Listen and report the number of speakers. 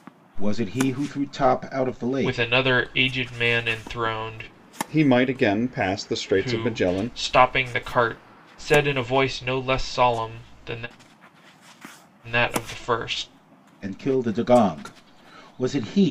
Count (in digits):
3